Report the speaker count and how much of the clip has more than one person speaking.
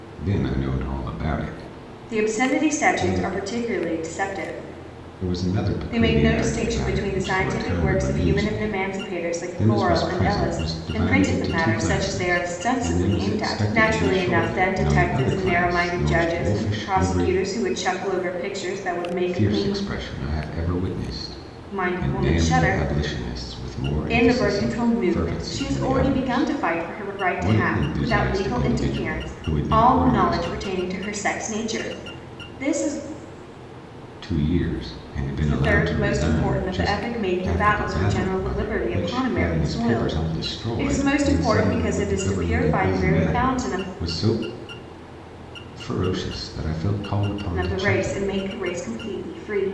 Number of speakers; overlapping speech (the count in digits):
2, about 57%